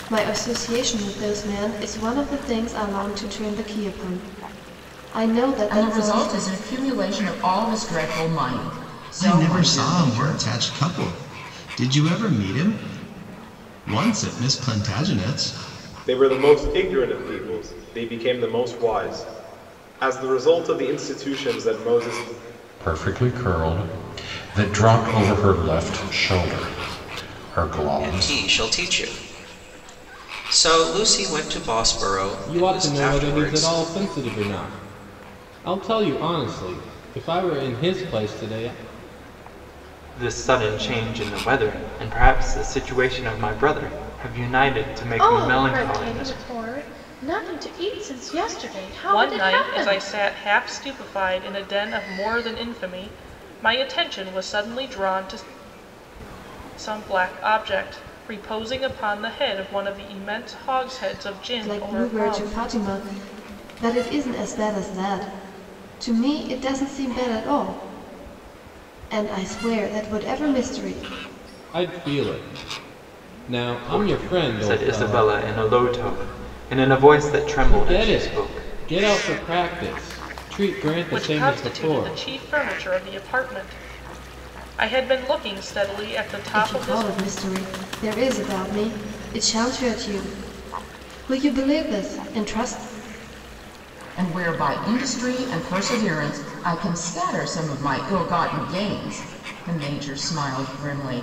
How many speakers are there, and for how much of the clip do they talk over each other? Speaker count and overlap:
ten, about 11%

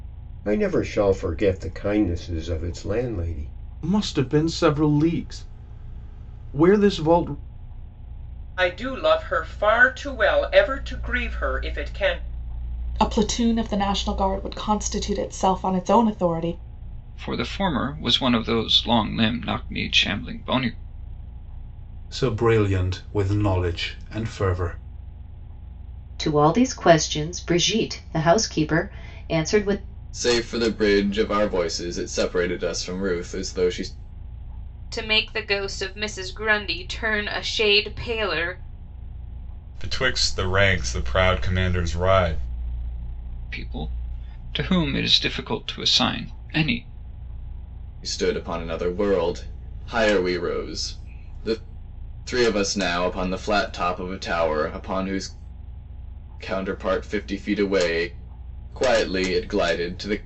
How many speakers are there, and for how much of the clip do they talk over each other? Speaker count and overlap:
ten, no overlap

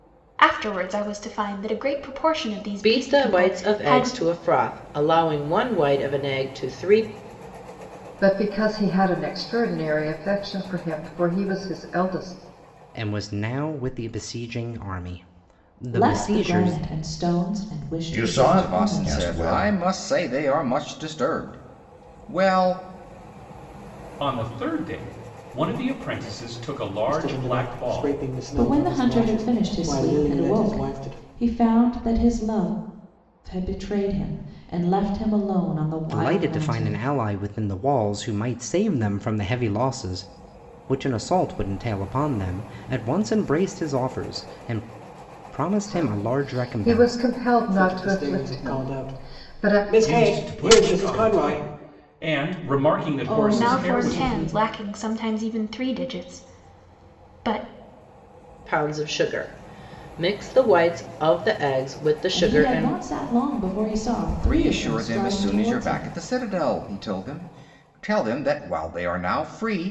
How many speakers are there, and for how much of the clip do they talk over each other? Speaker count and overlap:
nine, about 25%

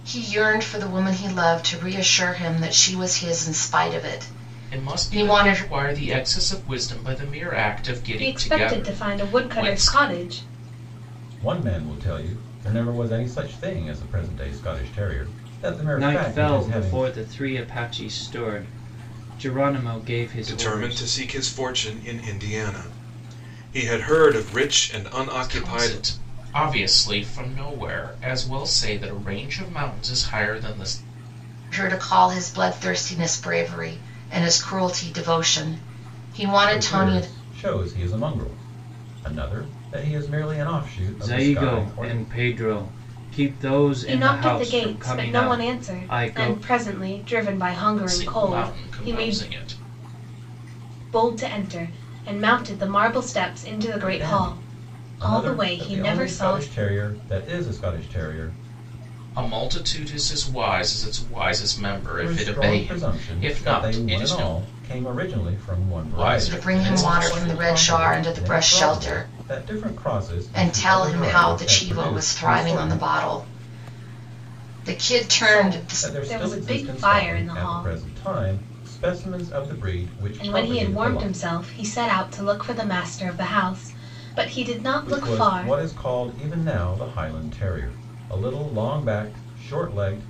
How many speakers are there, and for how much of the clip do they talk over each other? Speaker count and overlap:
six, about 29%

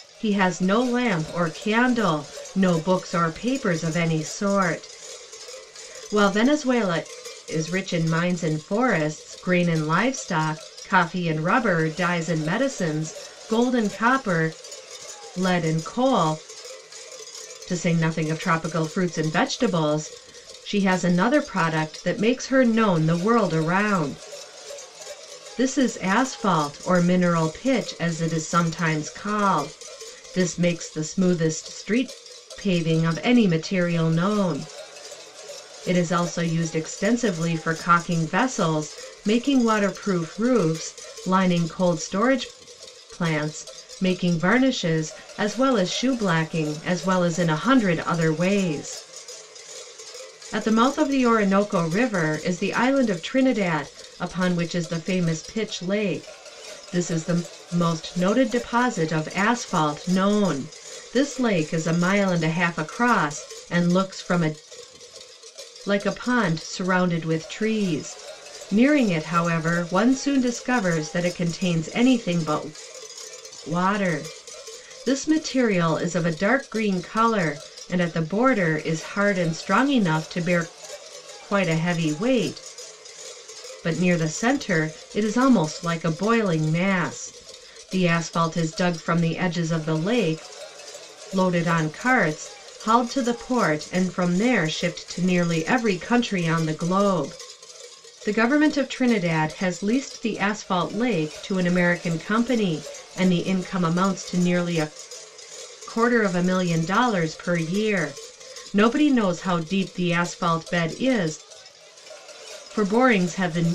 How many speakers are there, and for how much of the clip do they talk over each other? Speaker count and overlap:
one, no overlap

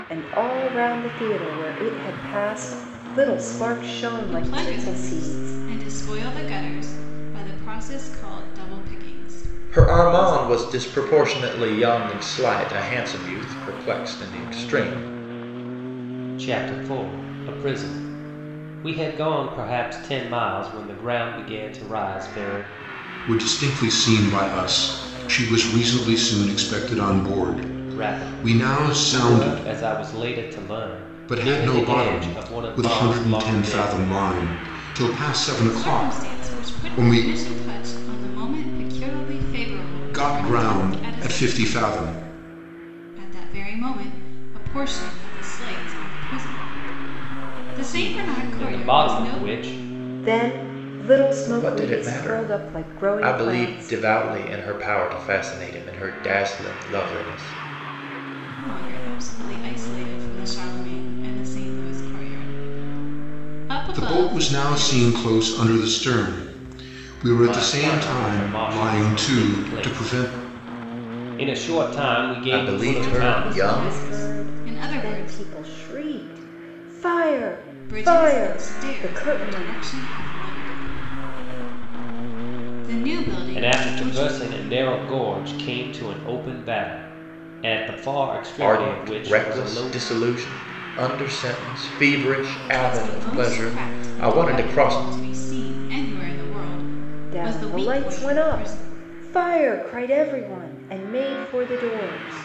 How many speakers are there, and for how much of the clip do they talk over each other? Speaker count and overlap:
five, about 29%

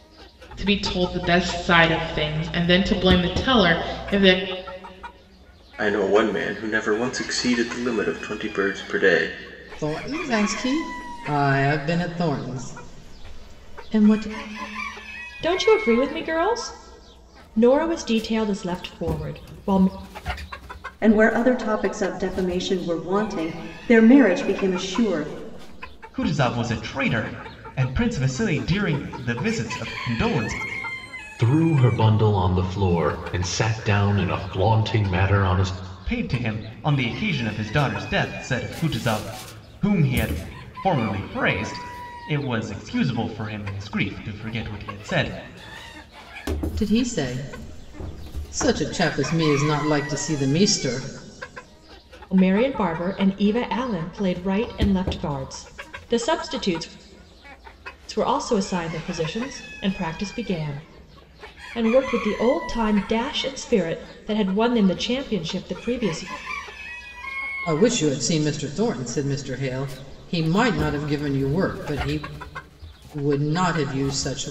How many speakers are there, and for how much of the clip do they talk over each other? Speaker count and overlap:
seven, no overlap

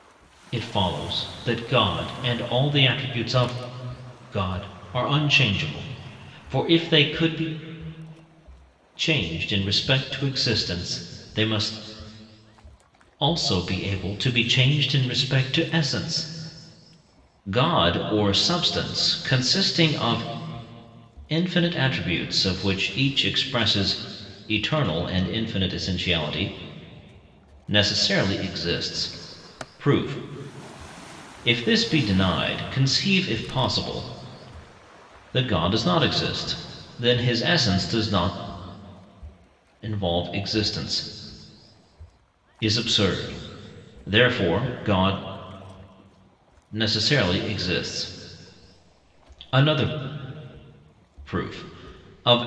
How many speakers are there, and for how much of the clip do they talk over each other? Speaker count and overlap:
one, no overlap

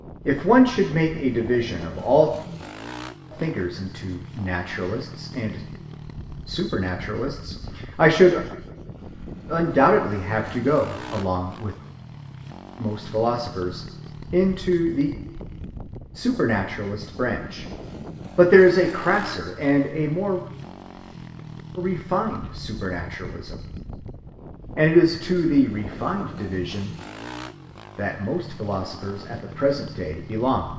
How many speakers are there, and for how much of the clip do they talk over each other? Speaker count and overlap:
one, no overlap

